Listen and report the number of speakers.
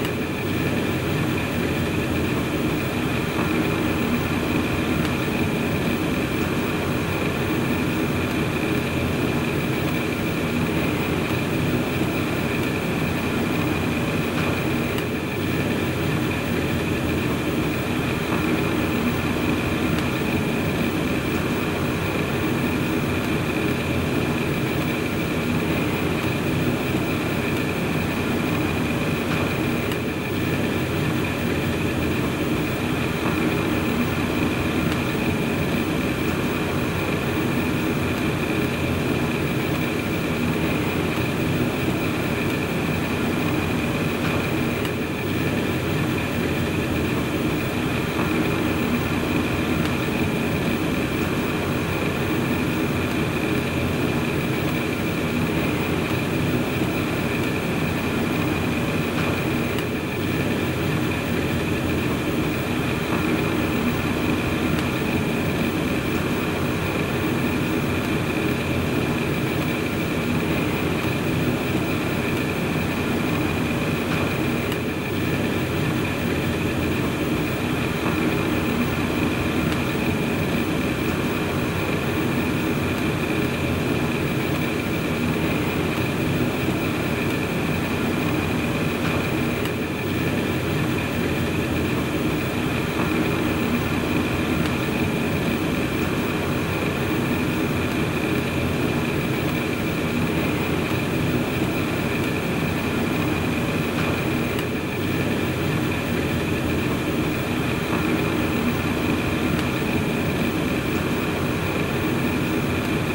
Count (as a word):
zero